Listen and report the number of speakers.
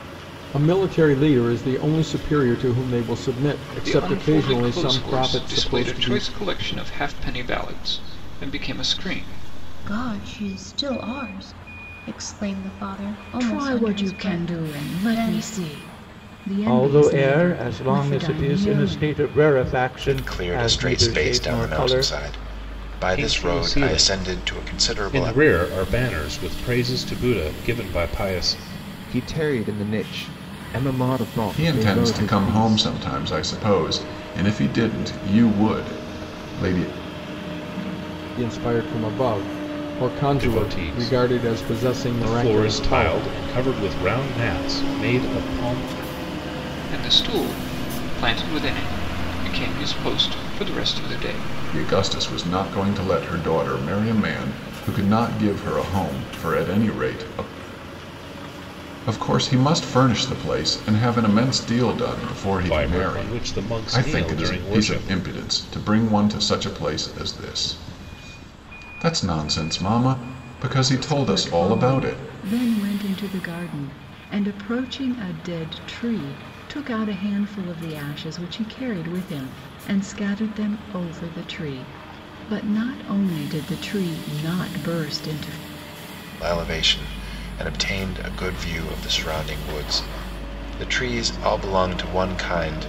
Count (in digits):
9